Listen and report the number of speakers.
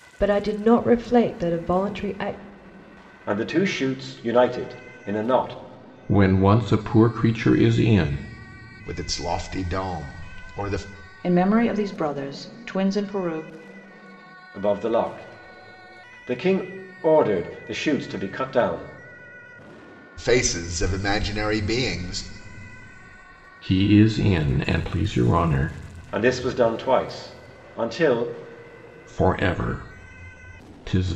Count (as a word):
five